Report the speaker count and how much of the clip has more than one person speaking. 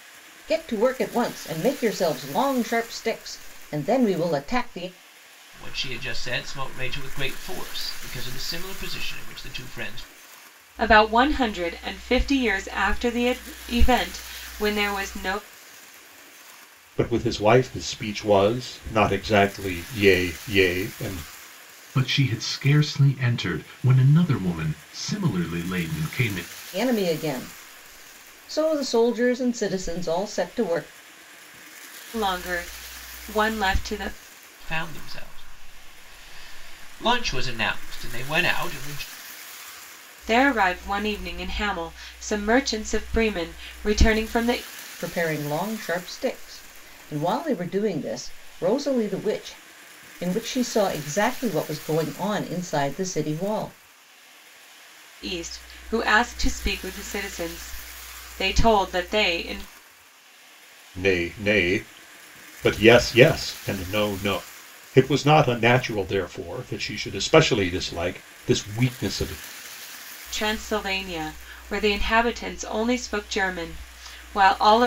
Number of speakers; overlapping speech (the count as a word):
five, no overlap